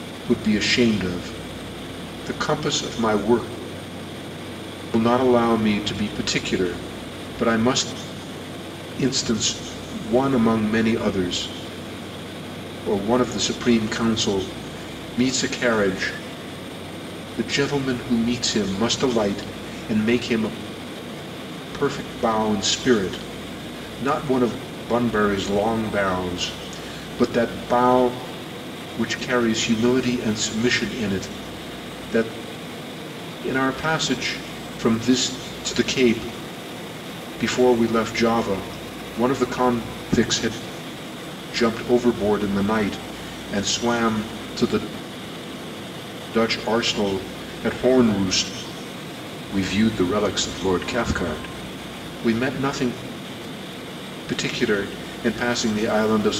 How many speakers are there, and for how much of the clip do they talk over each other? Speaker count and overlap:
one, no overlap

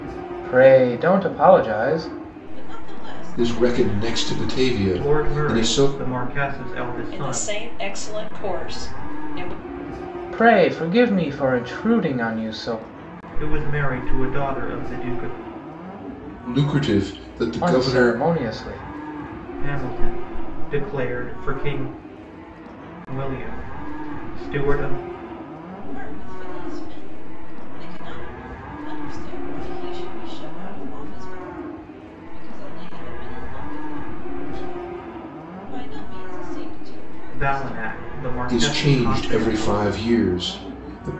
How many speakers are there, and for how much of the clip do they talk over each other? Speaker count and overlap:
five, about 13%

